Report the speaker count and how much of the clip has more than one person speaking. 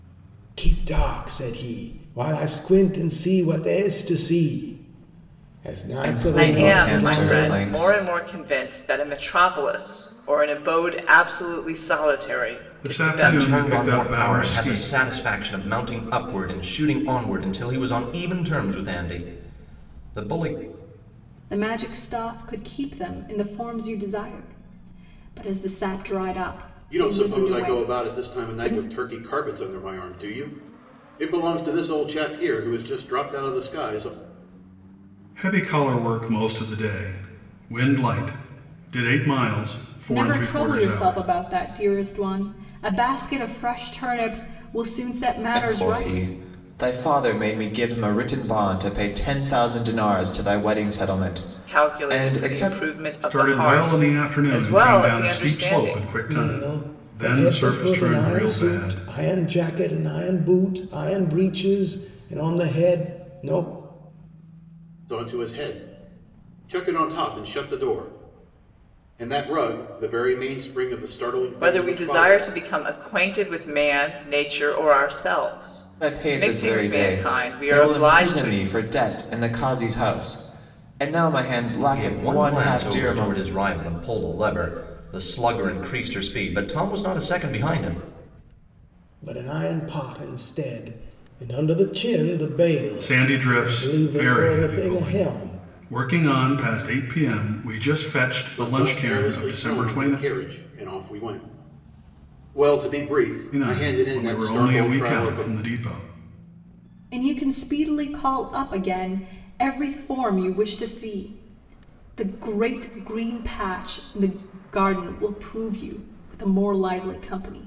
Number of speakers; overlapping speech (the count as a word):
seven, about 22%